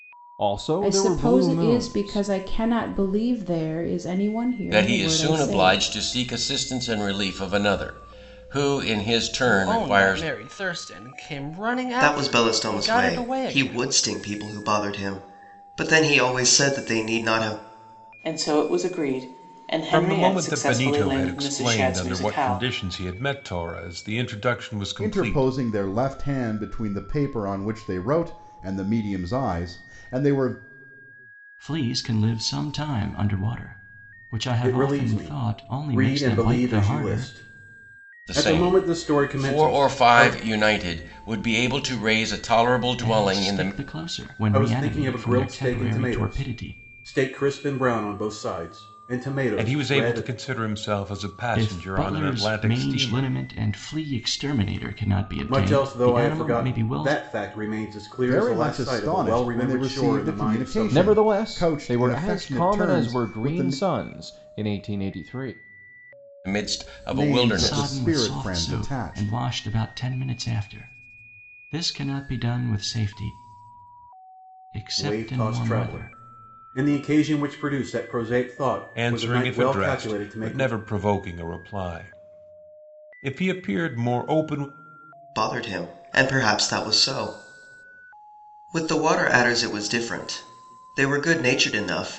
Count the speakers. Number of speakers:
ten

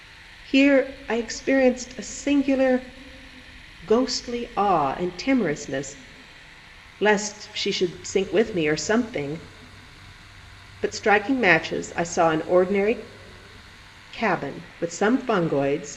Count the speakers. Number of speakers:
one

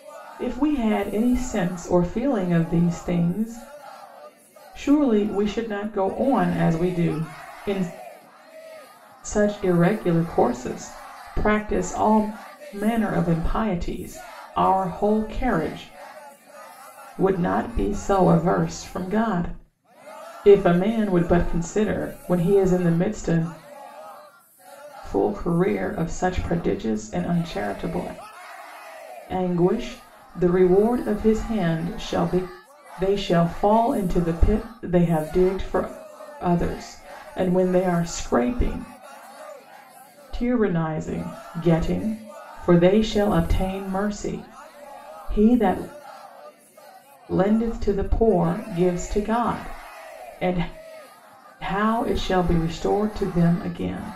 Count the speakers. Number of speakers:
one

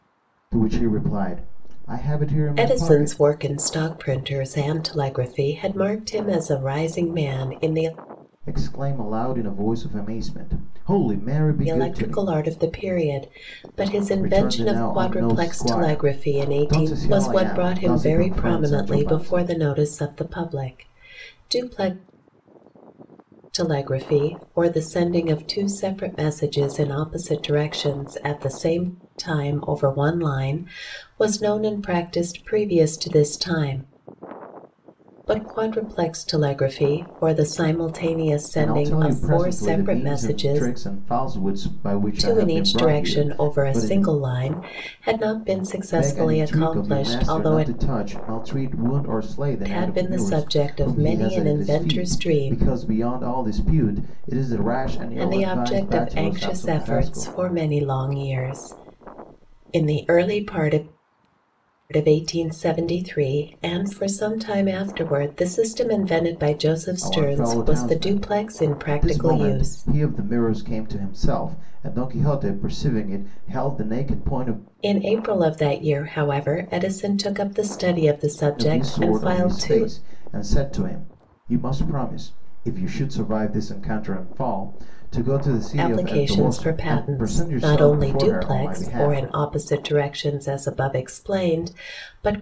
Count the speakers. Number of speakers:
two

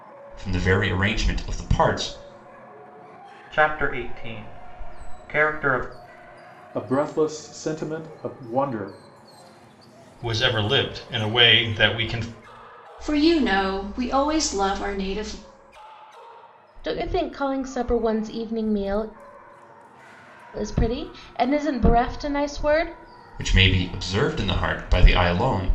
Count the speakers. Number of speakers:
six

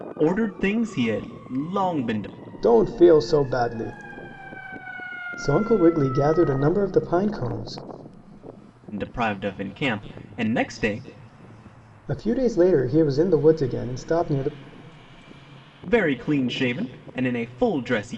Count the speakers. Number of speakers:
two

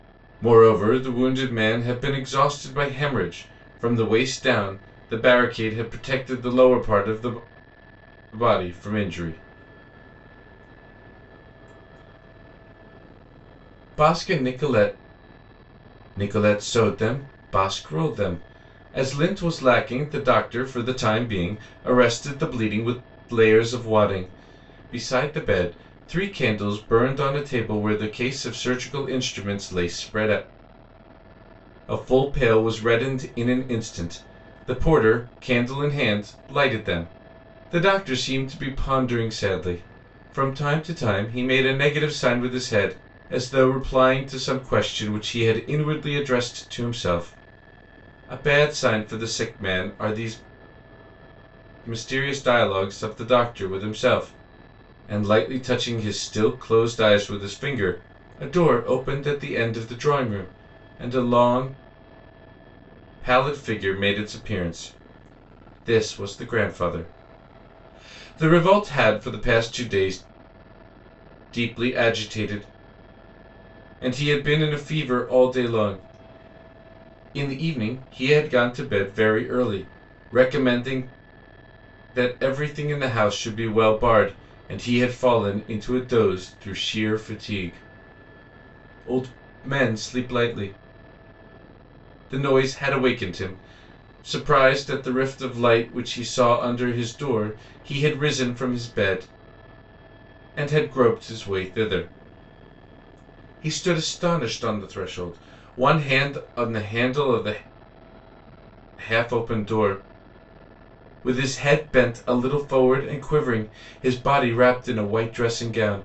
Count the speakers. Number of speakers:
one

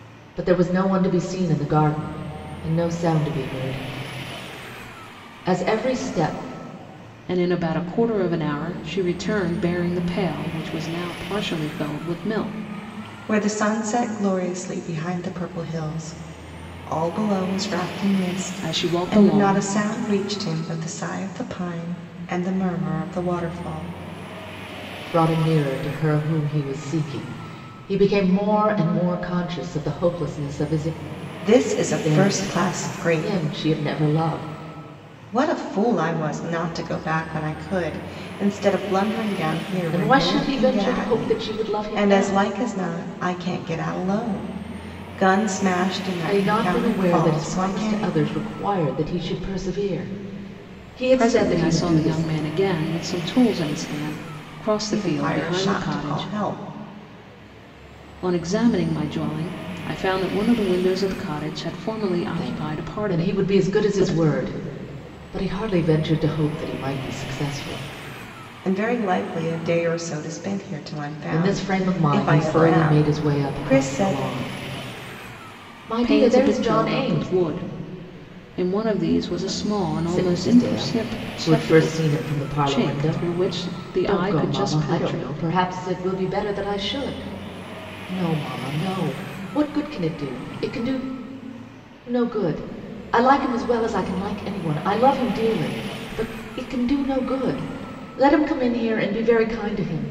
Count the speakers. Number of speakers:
three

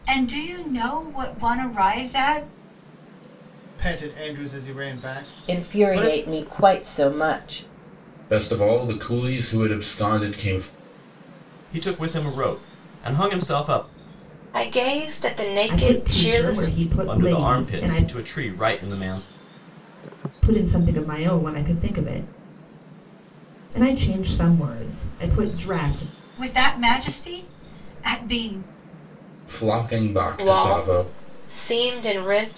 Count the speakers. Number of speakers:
seven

